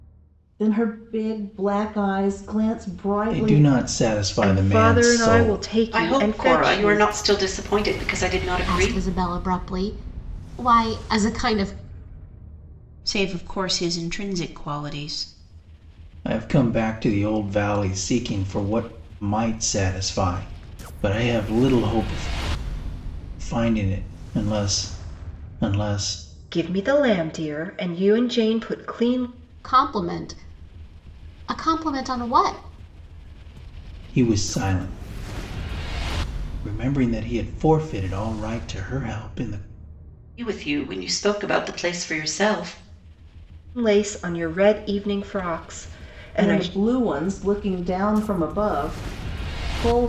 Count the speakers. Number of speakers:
6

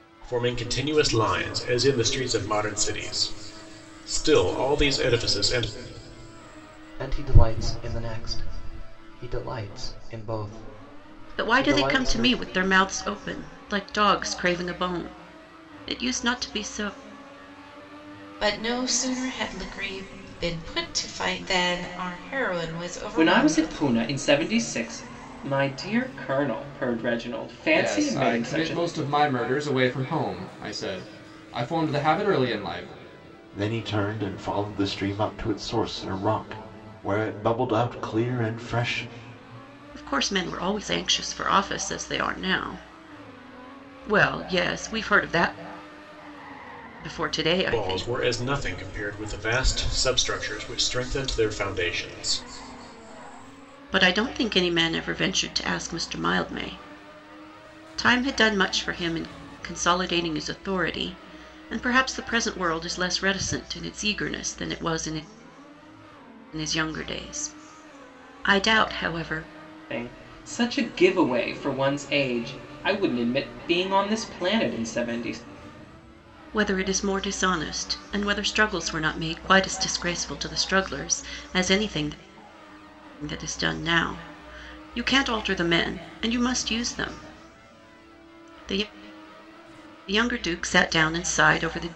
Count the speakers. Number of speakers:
7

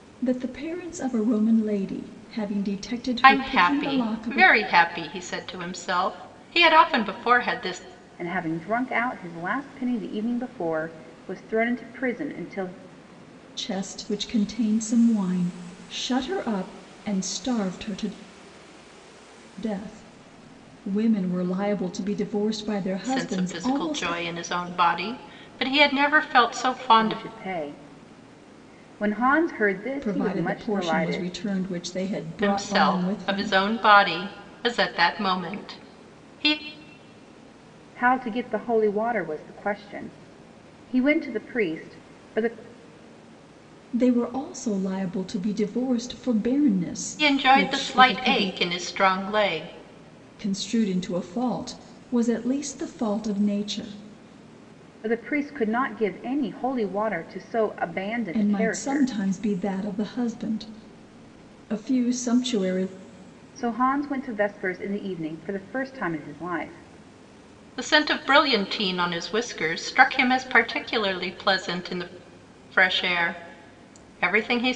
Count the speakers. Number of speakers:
3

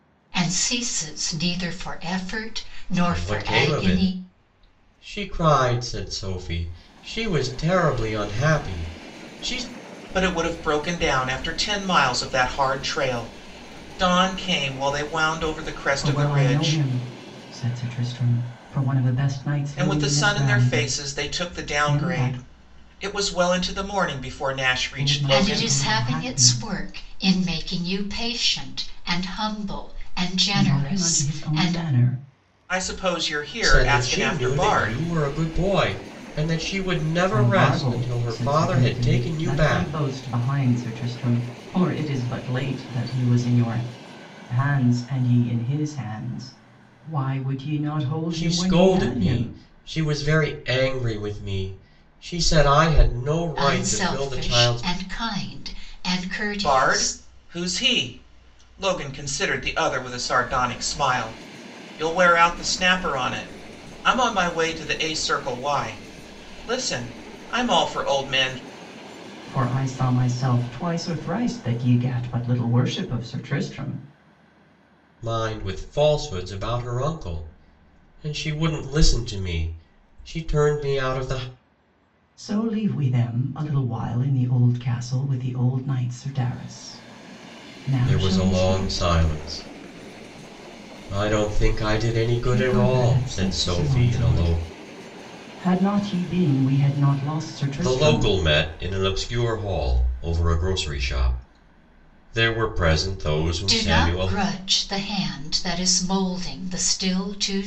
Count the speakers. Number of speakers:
4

